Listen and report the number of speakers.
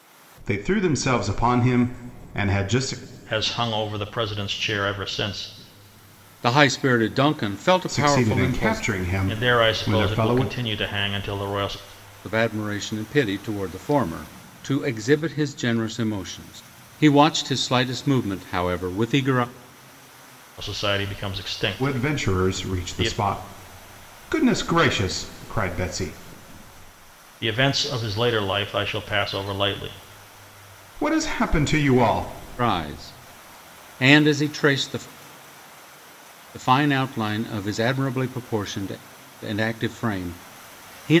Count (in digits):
3